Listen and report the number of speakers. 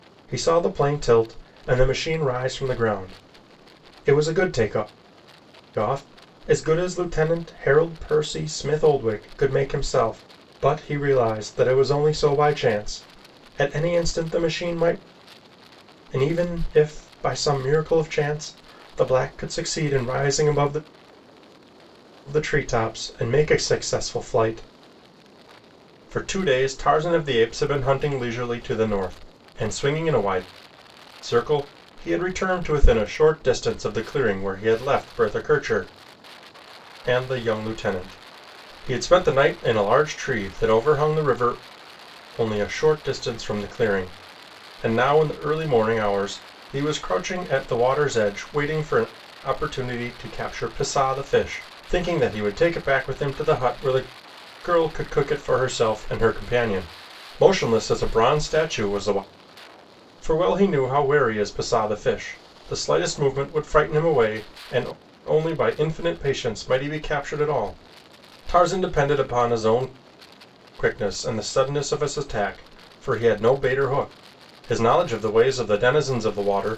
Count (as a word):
one